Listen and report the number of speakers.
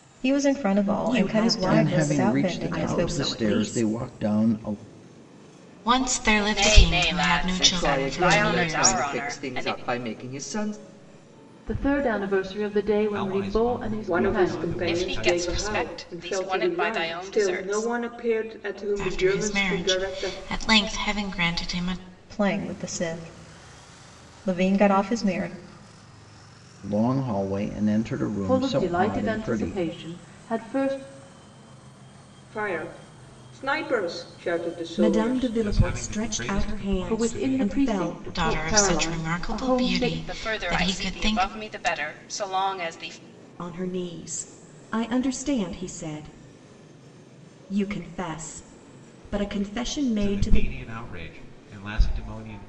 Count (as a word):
nine